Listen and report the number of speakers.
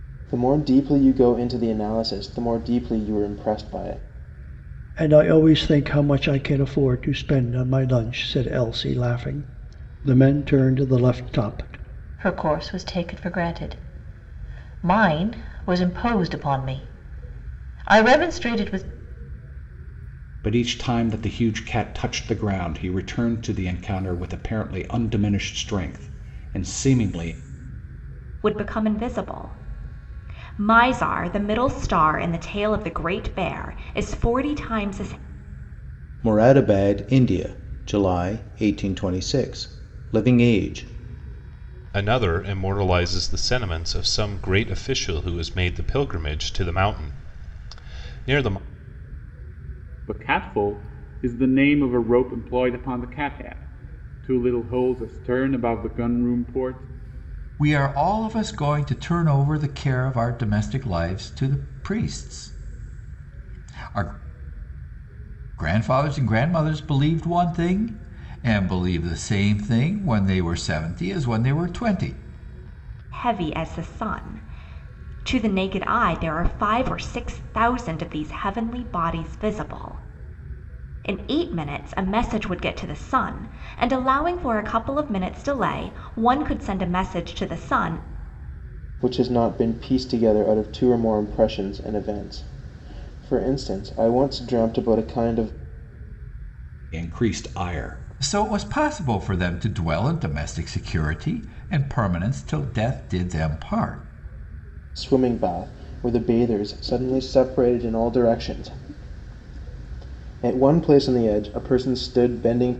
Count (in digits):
9